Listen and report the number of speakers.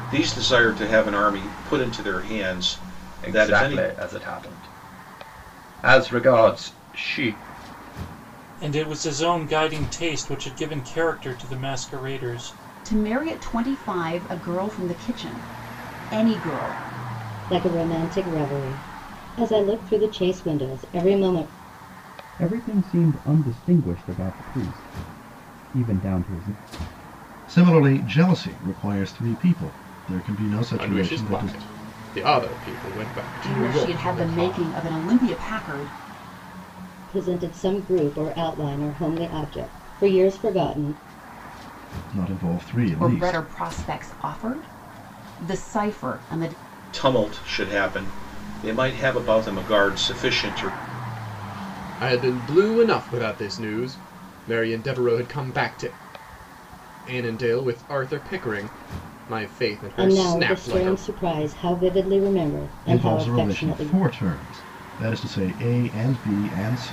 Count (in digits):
8